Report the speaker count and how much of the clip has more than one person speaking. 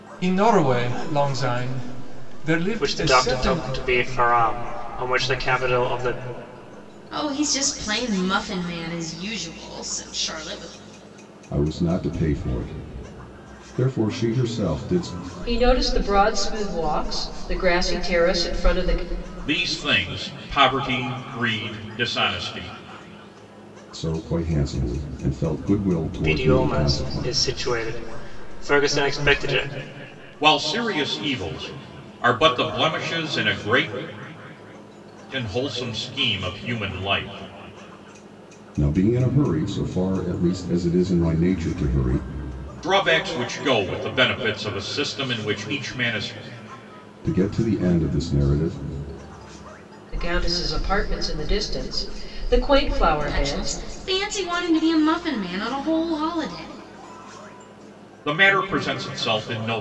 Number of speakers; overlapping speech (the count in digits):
6, about 5%